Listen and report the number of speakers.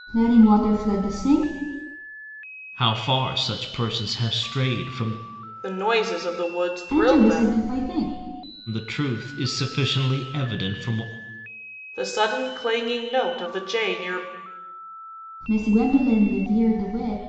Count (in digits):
3